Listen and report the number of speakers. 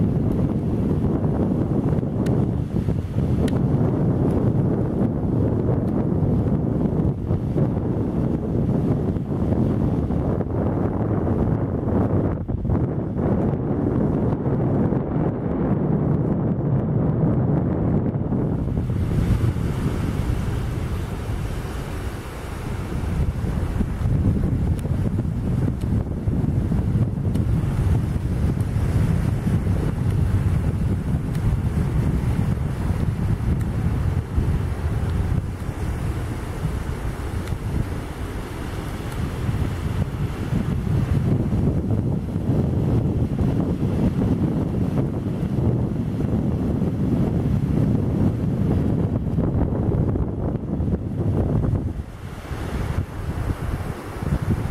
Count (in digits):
0